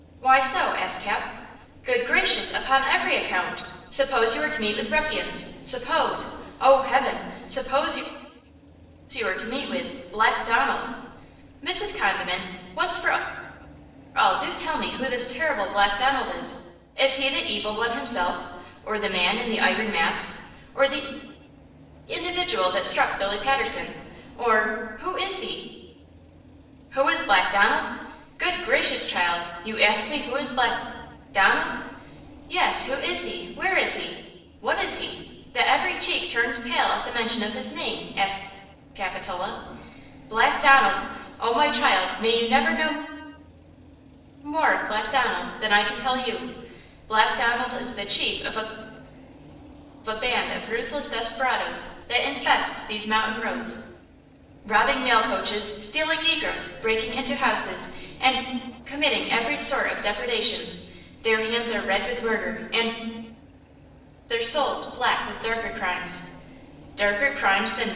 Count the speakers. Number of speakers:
1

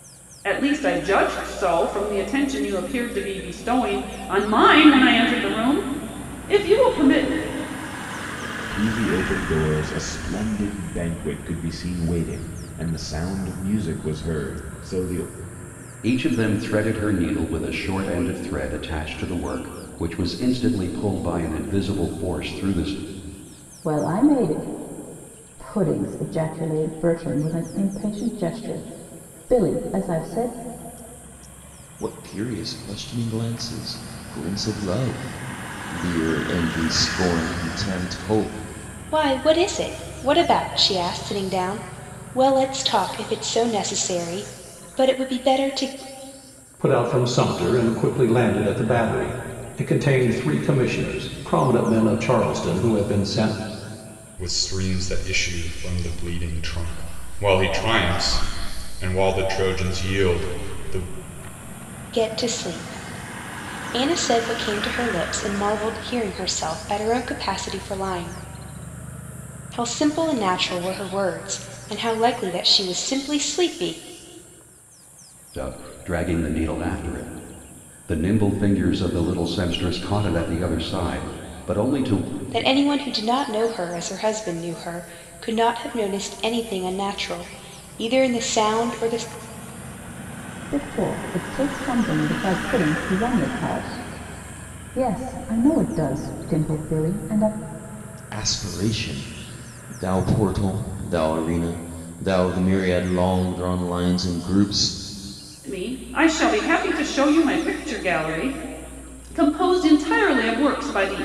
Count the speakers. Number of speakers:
8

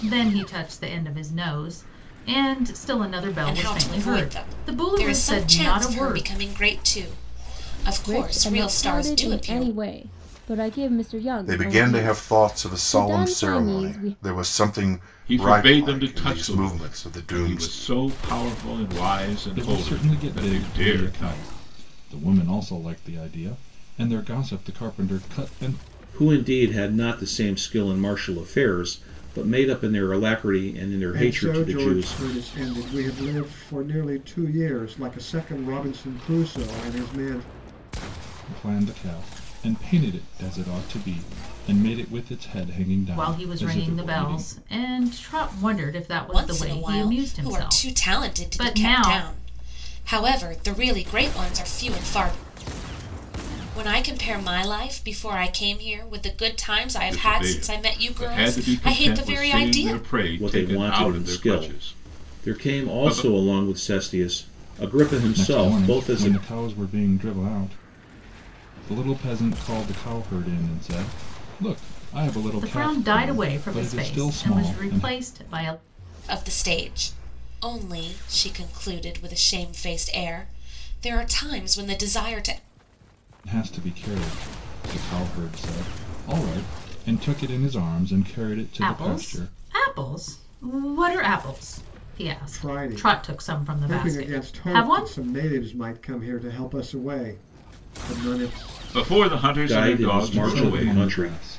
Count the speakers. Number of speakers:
8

